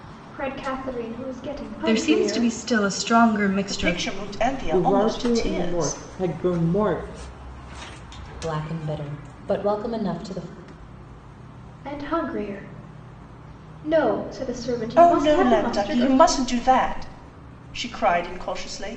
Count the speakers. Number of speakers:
5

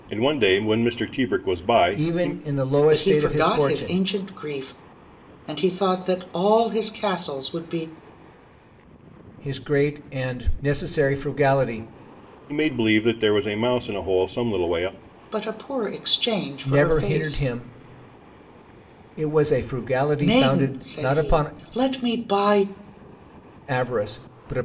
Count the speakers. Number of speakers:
3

